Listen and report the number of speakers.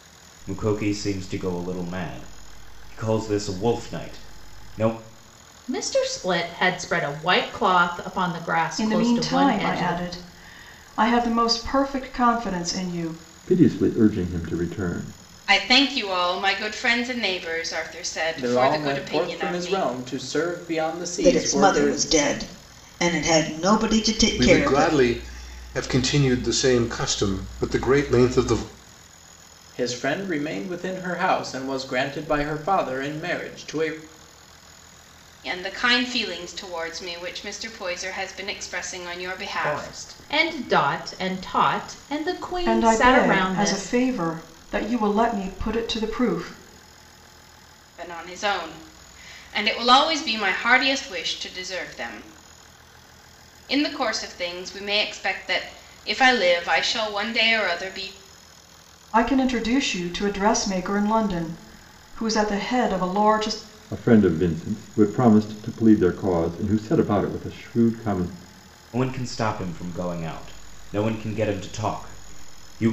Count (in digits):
8